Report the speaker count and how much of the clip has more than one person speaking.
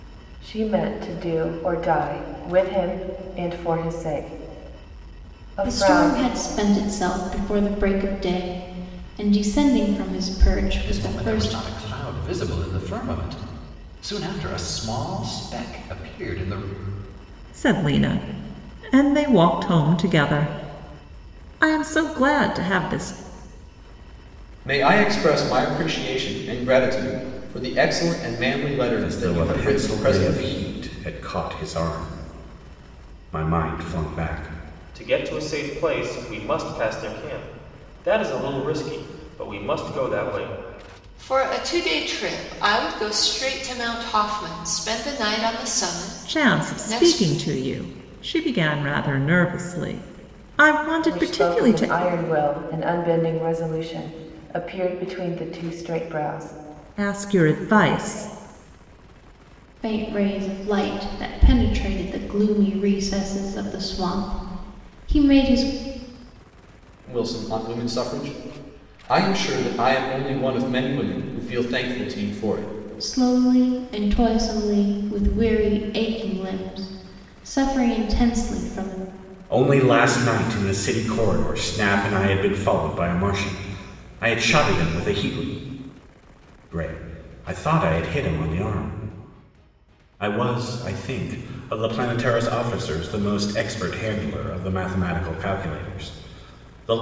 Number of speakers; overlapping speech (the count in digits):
8, about 5%